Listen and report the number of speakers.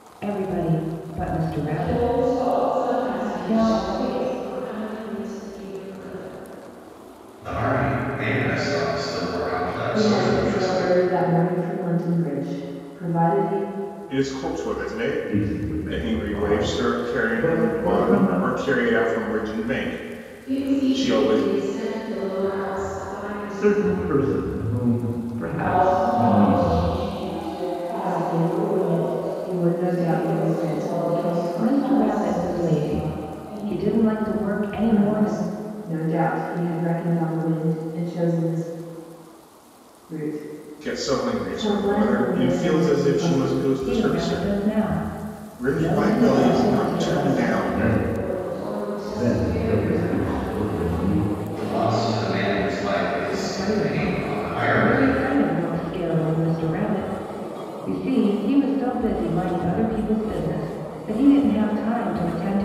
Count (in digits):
7